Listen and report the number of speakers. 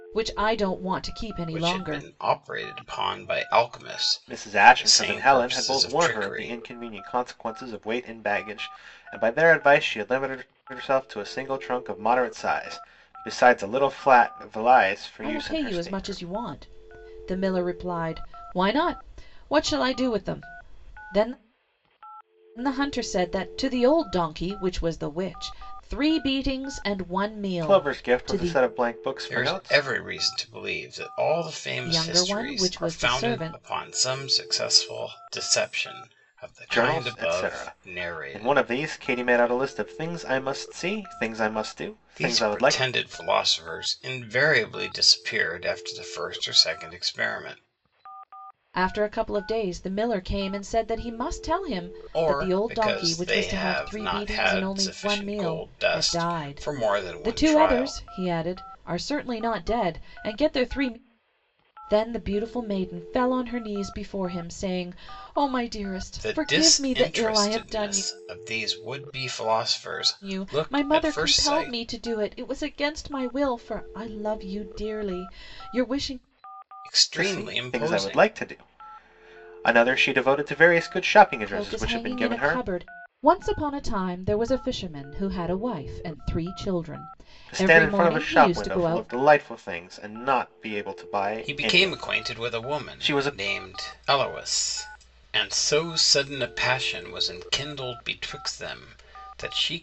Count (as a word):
three